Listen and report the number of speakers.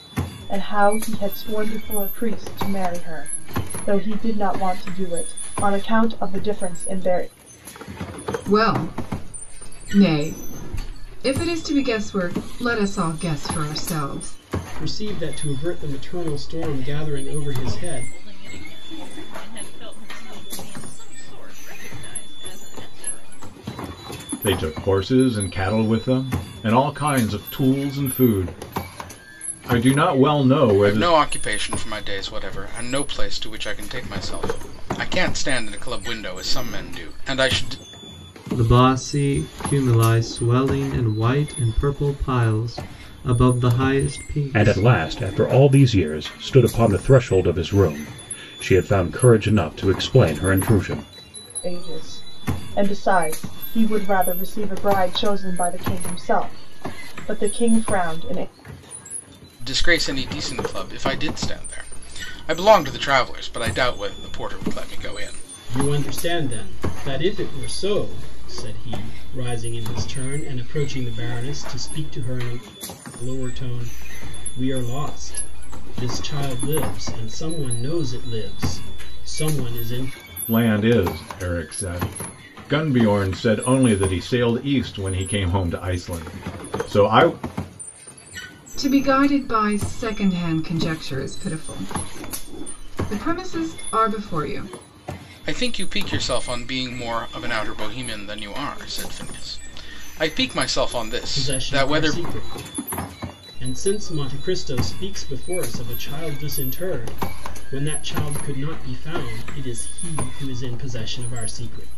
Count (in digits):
8